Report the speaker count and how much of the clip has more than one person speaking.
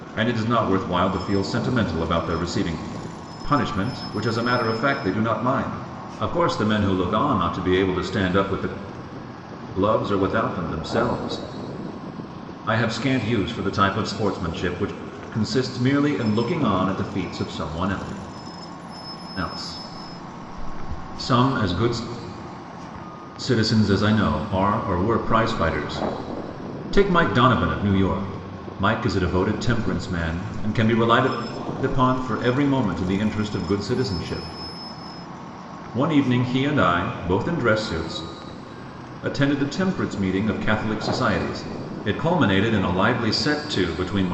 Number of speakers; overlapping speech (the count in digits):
1, no overlap